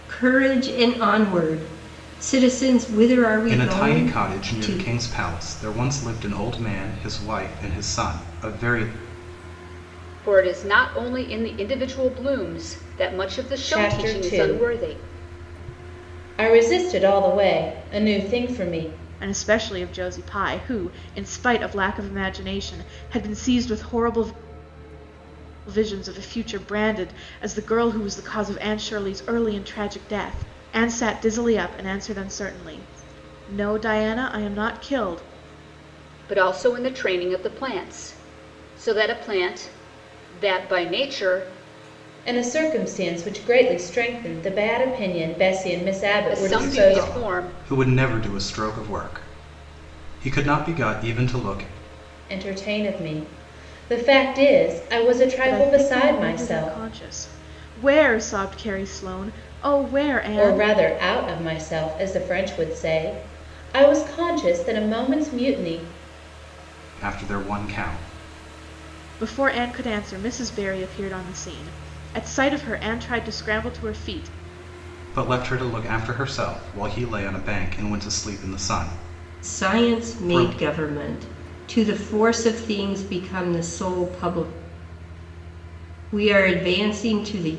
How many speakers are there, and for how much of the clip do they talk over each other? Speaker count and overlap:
5, about 8%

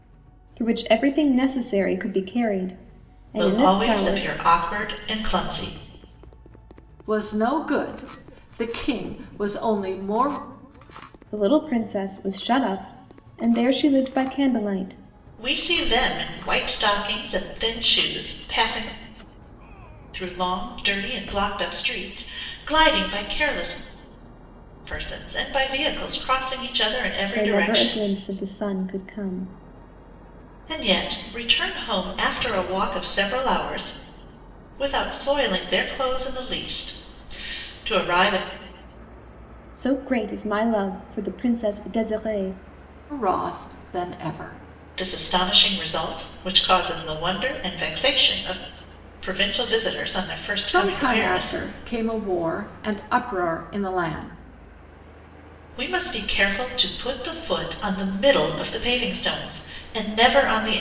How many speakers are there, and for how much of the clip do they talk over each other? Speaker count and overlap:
3, about 4%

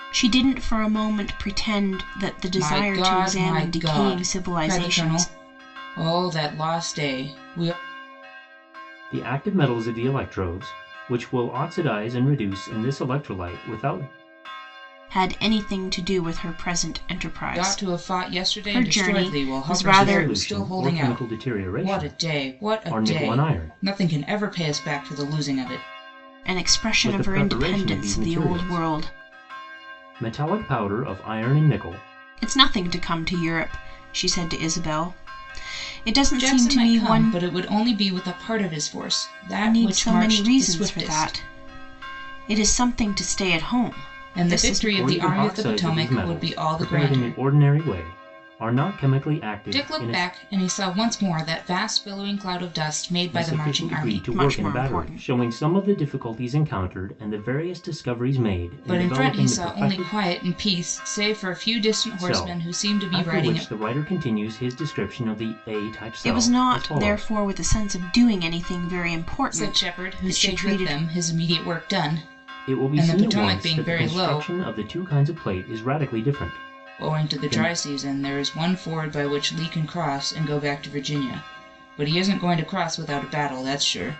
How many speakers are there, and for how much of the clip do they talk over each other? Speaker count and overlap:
3, about 33%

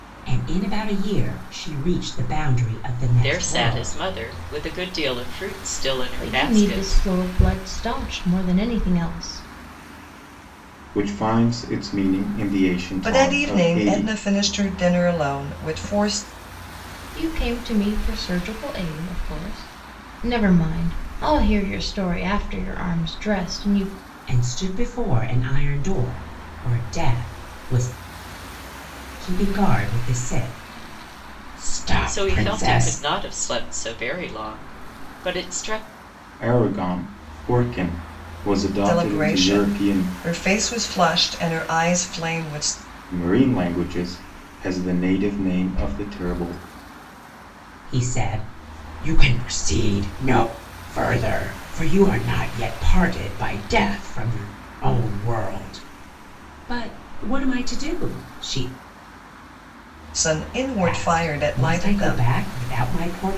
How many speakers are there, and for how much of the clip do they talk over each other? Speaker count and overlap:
5, about 10%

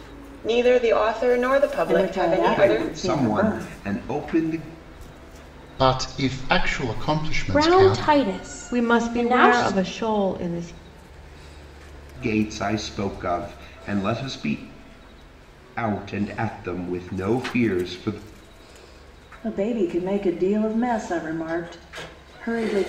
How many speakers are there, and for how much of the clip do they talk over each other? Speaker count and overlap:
6, about 16%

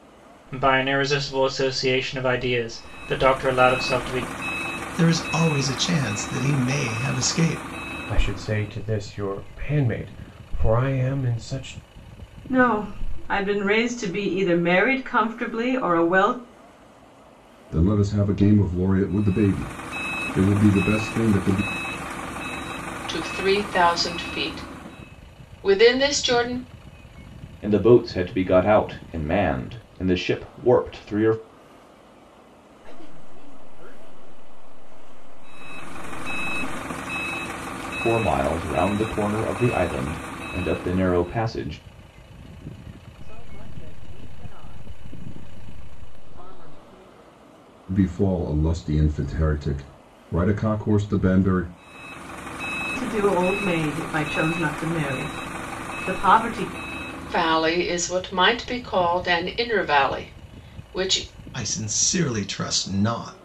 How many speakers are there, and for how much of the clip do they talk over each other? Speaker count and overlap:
8, no overlap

